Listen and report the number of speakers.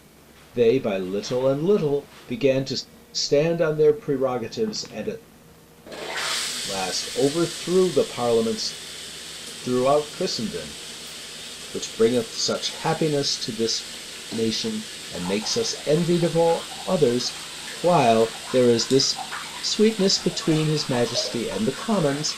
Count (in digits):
1